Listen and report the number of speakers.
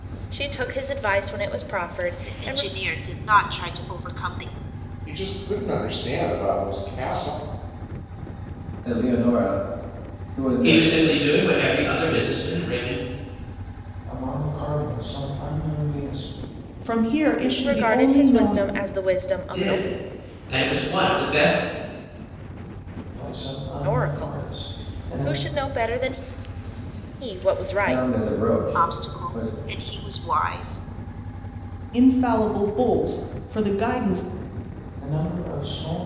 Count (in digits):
7